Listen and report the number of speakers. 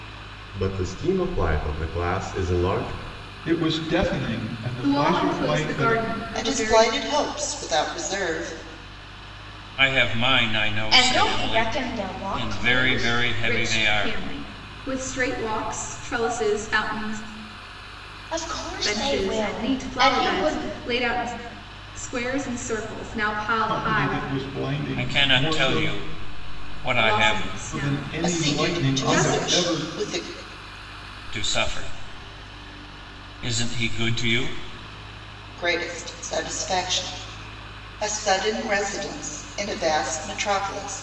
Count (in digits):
6